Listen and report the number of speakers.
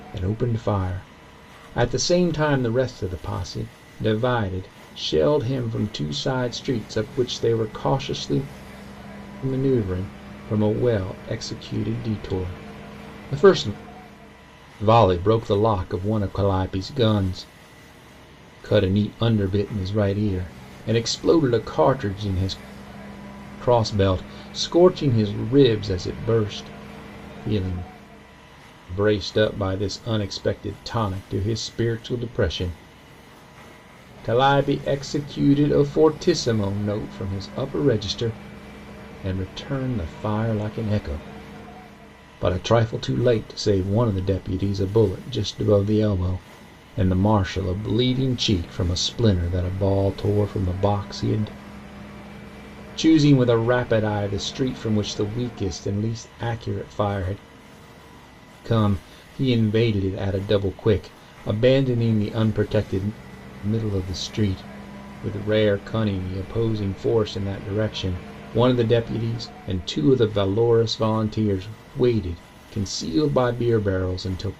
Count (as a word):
one